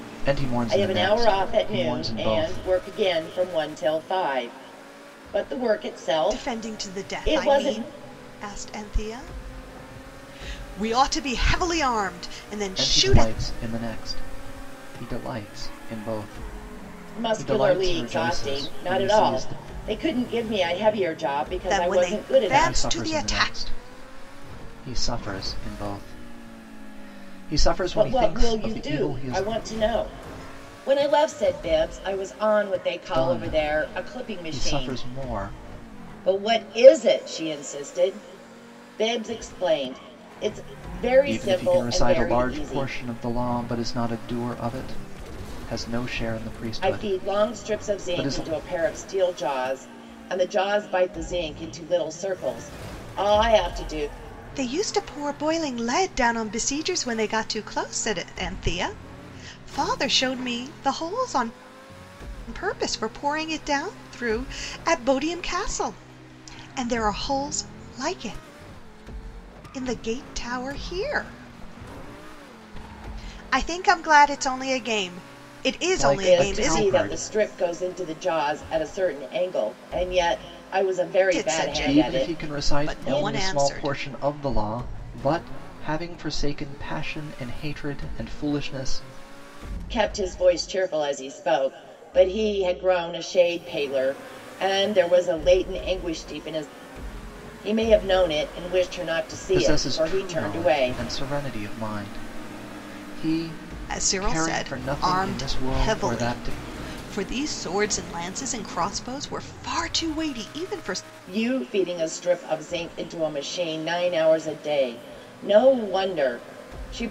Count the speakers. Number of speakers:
three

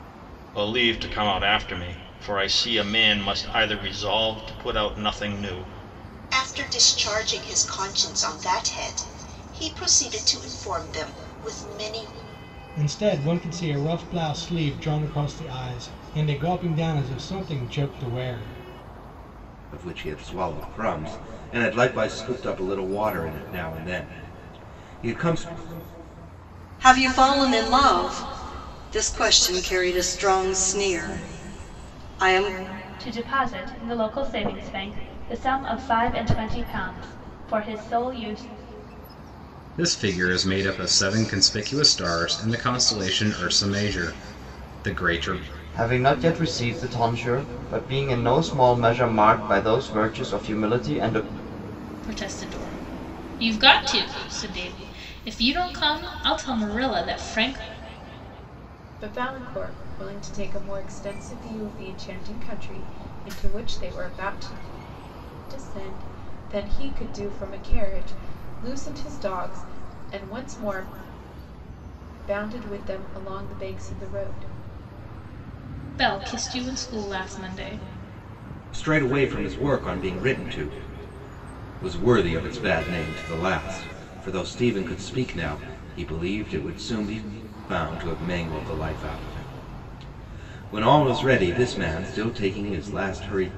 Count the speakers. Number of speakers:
ten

